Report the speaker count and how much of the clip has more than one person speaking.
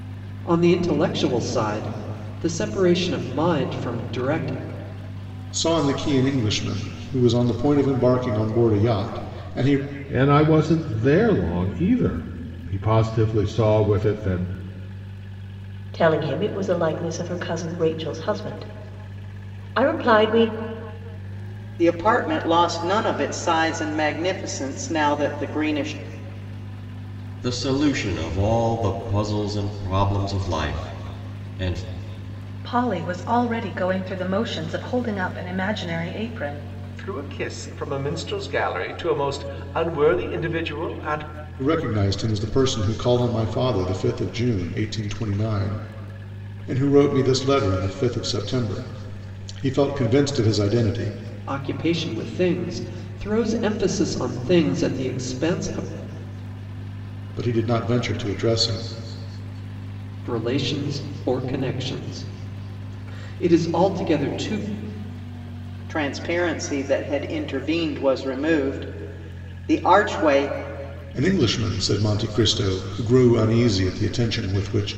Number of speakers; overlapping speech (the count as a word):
eight, no overlap